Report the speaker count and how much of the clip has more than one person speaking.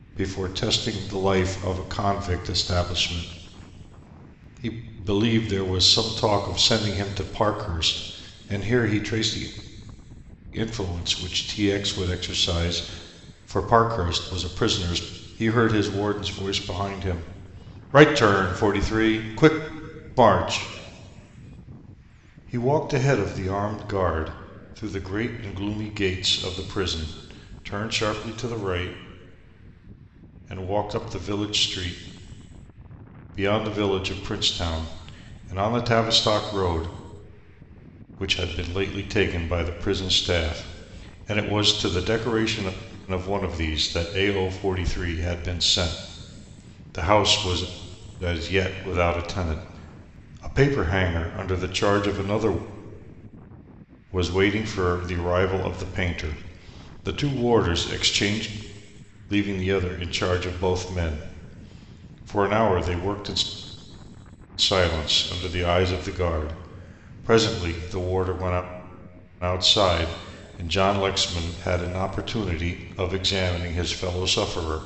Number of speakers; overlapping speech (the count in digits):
1, no overlap